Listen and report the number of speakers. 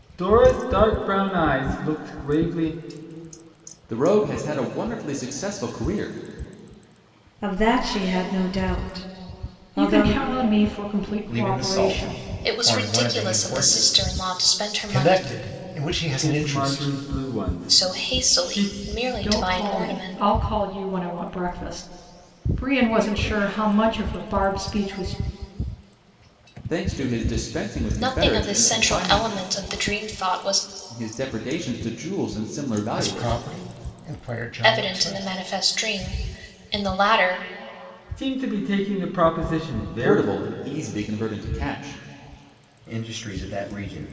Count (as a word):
seven